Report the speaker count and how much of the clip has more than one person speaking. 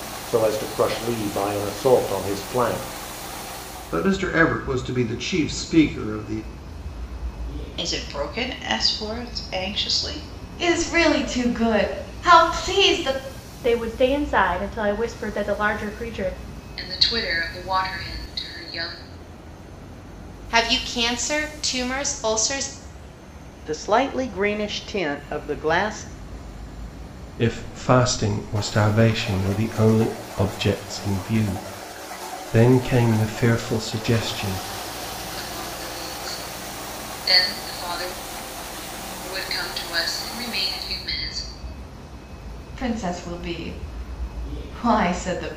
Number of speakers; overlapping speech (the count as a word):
nine, no overlap